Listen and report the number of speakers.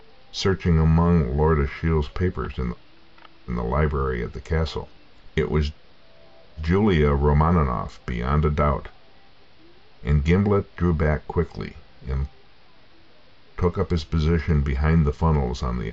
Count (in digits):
1